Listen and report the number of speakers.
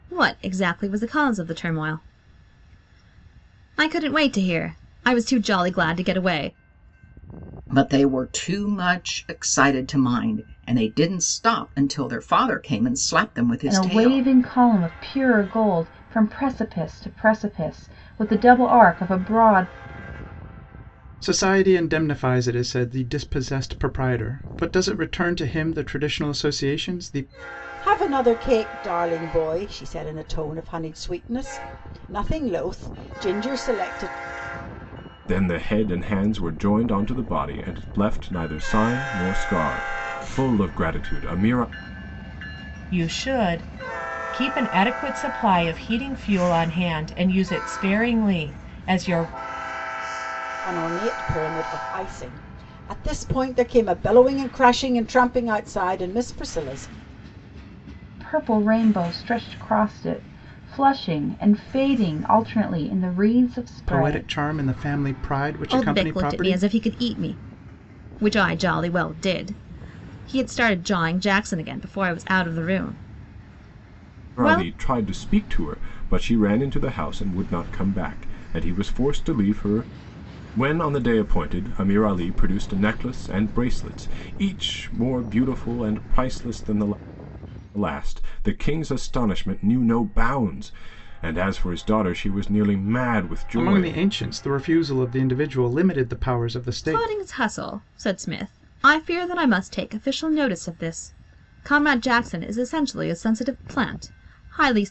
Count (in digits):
7